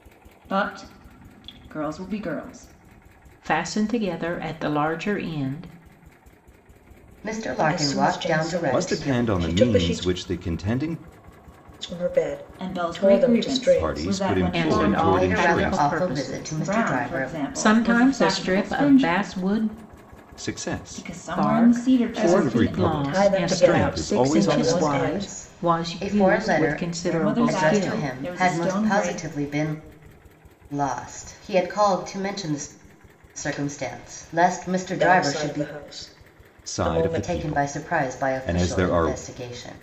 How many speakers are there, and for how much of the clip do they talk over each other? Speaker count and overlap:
5, about 51%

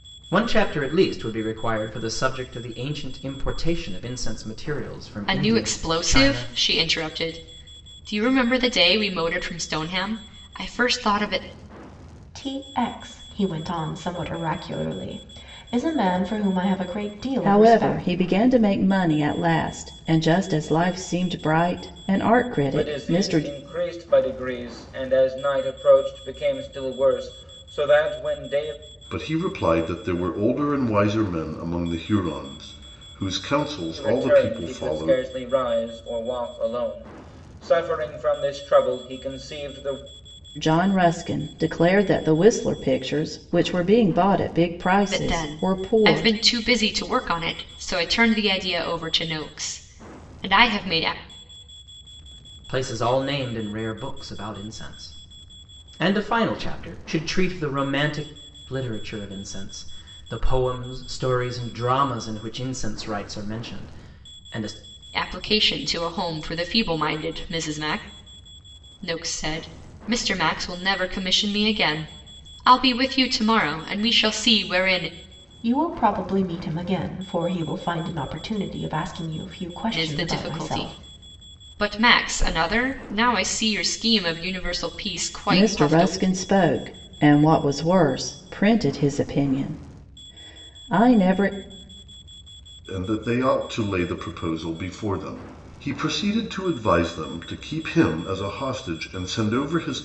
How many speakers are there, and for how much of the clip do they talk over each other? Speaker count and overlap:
6, about 7%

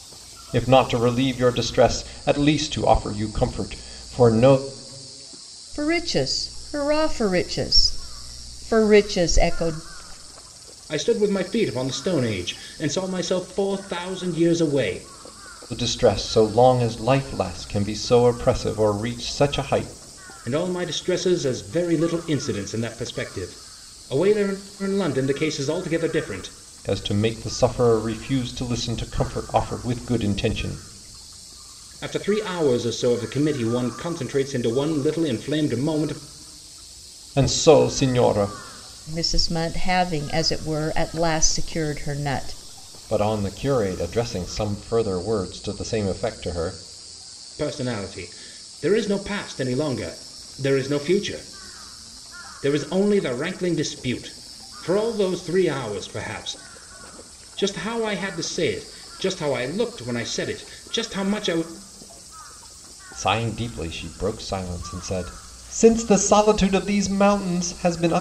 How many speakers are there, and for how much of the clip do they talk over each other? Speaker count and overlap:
3, no overlap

